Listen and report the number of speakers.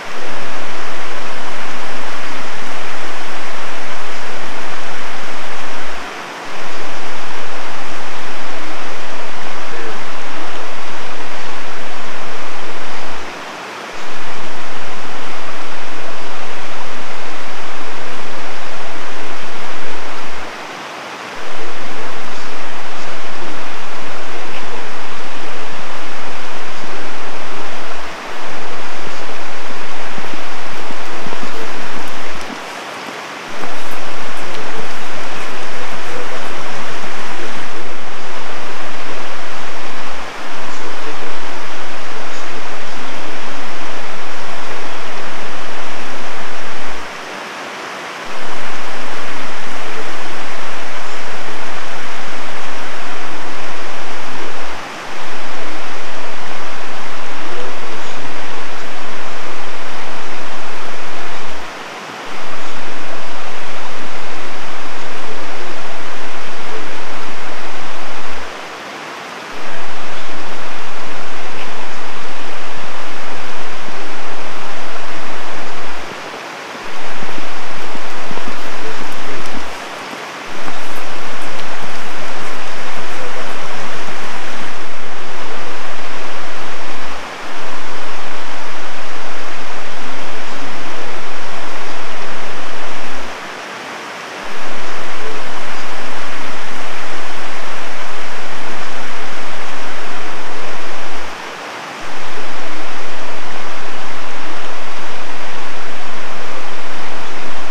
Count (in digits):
1